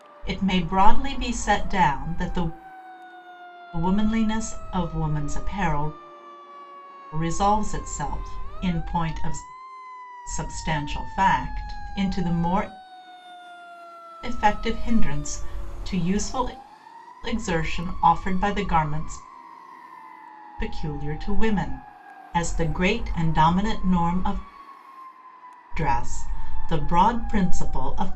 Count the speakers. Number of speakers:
1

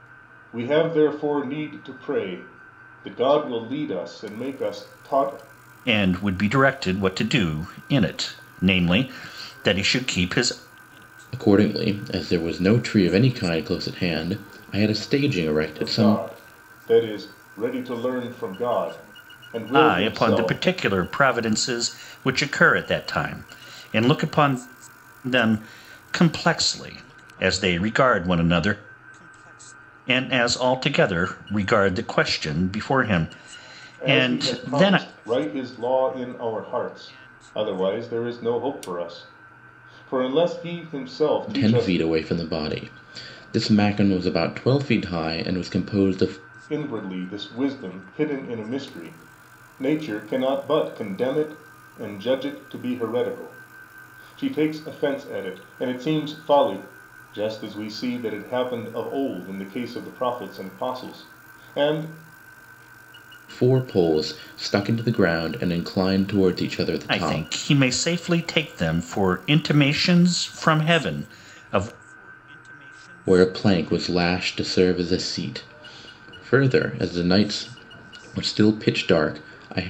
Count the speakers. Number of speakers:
3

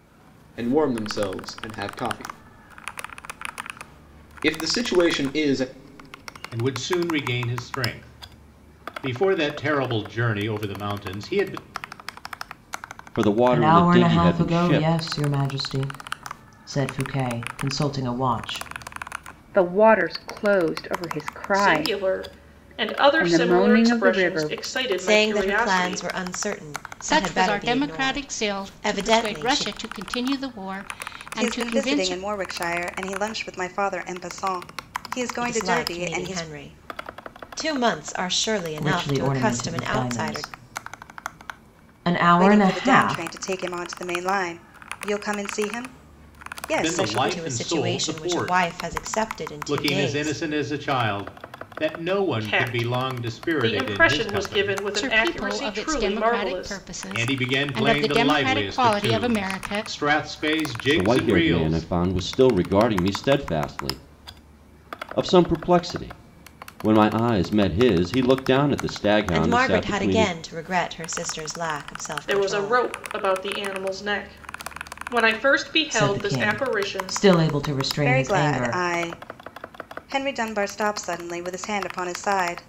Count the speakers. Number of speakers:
9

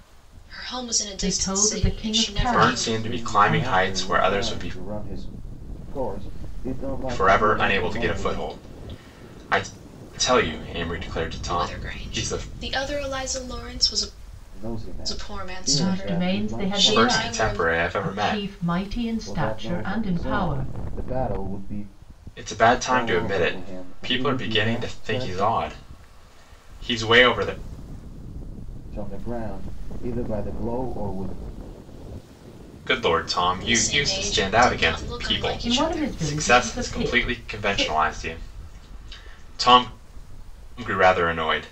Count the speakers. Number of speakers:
4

